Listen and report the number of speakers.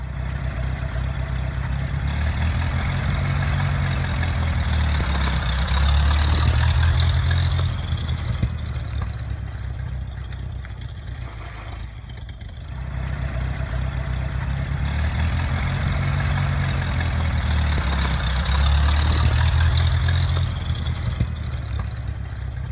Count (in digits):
0